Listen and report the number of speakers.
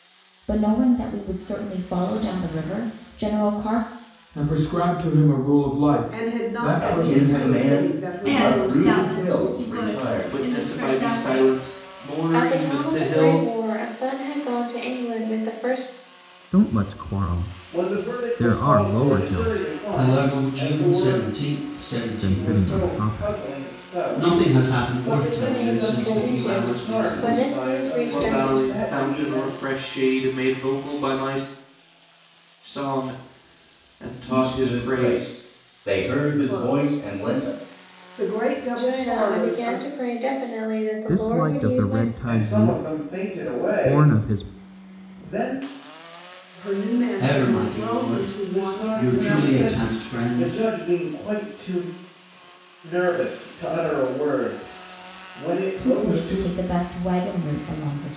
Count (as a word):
ten